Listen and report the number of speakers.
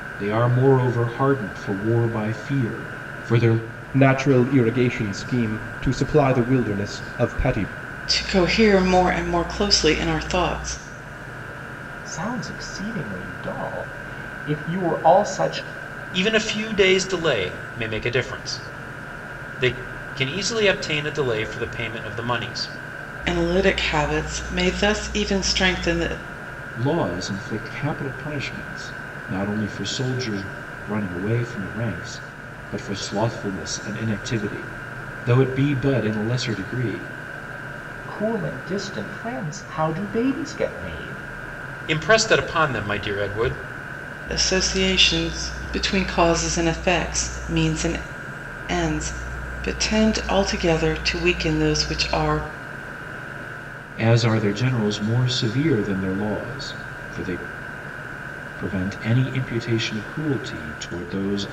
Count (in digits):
5